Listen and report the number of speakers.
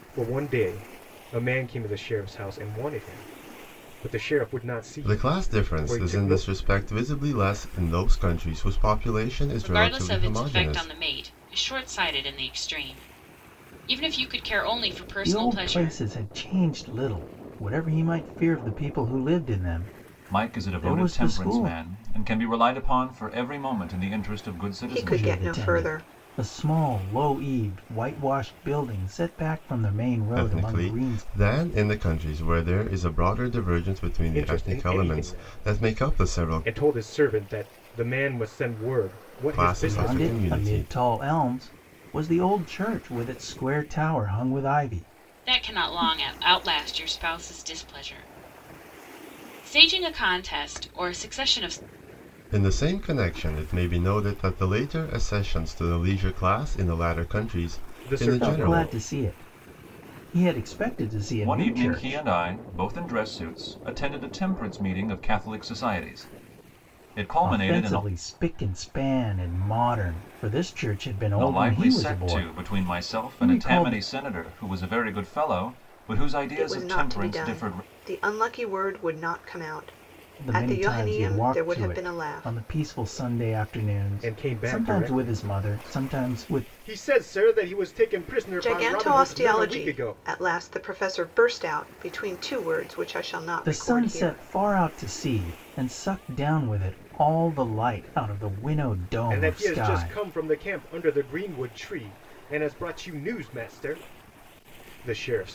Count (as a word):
six